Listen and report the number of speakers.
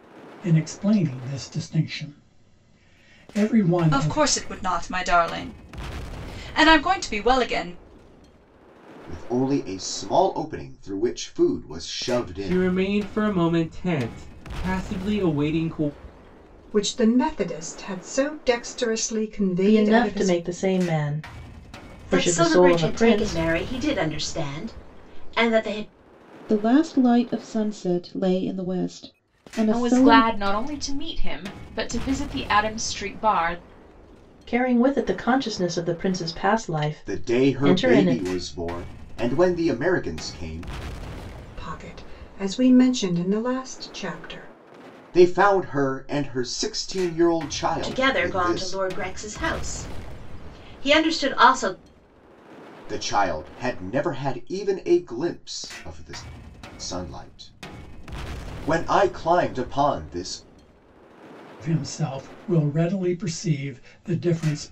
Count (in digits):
9